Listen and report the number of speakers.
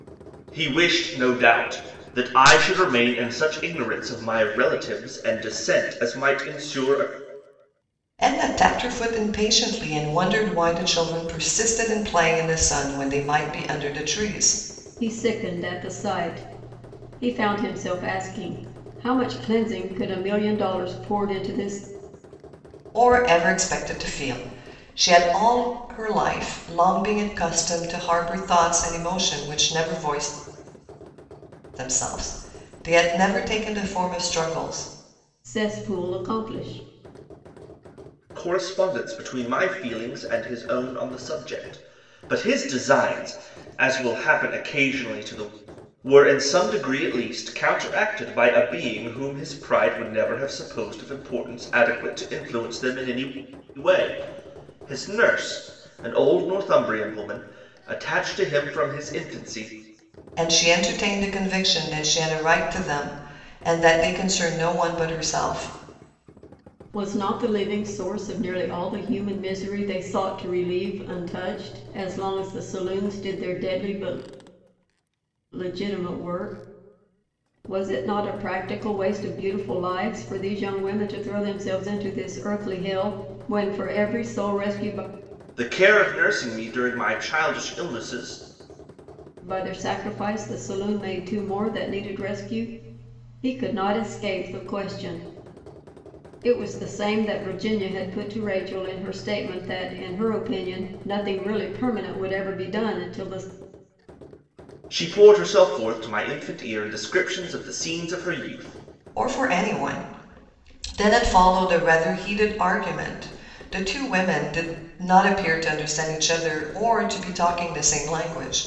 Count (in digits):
3